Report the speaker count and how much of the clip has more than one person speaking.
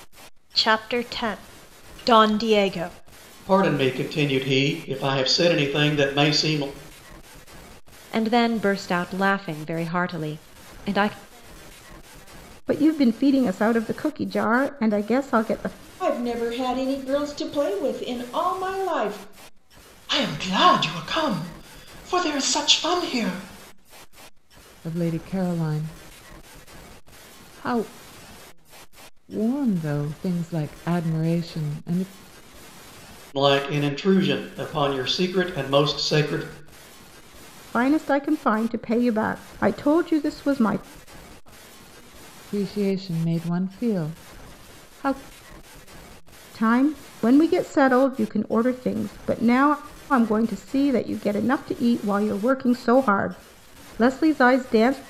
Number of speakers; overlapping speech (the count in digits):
7, no overlap